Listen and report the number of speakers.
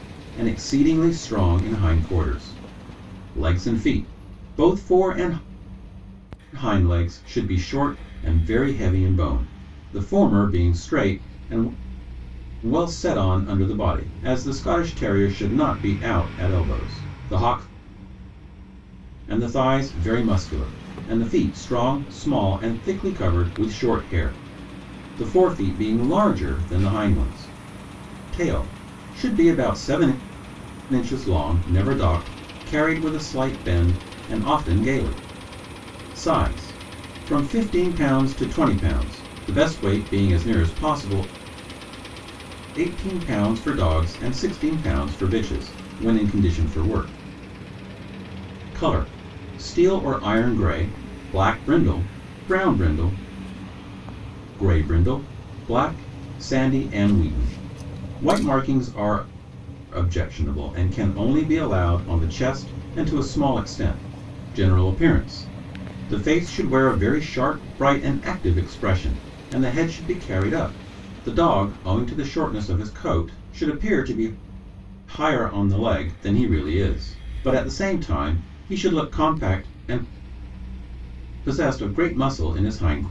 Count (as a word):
one